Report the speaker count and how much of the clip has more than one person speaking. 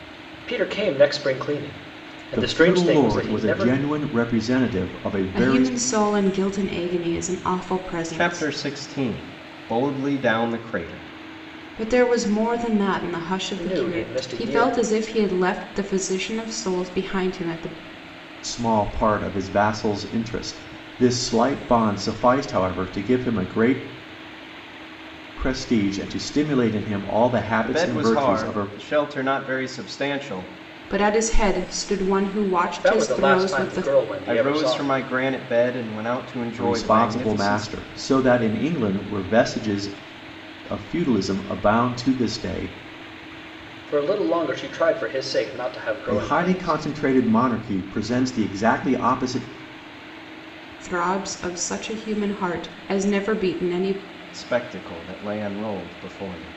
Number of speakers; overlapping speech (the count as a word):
four, about 15%